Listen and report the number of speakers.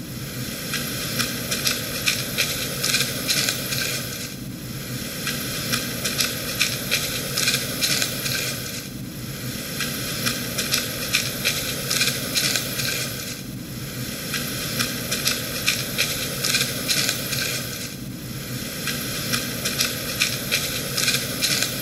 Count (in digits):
0